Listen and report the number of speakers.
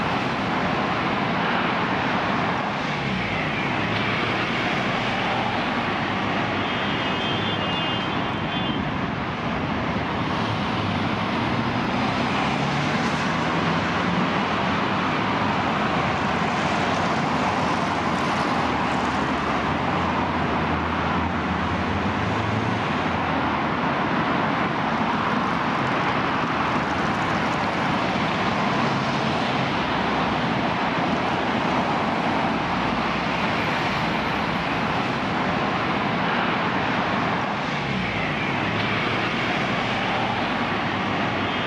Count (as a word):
zero